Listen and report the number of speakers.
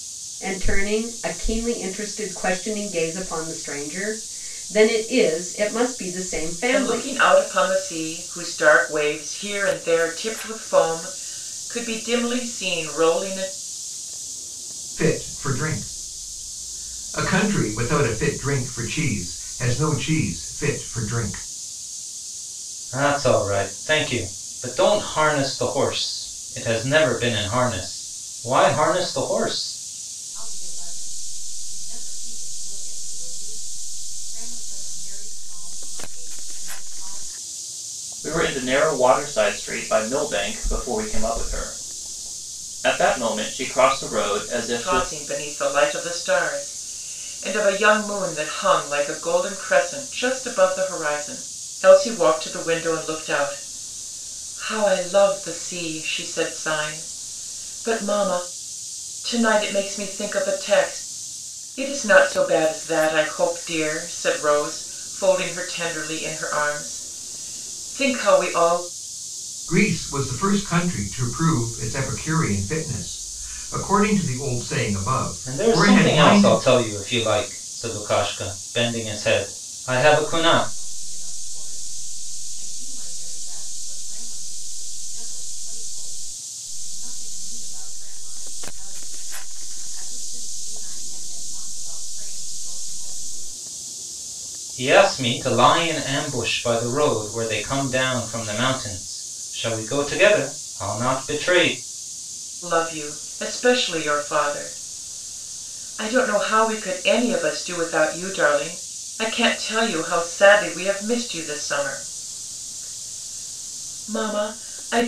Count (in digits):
6